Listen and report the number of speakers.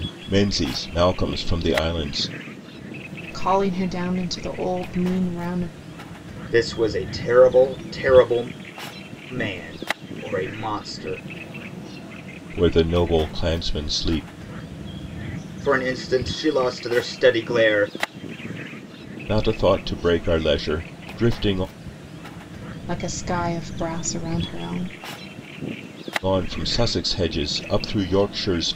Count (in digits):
3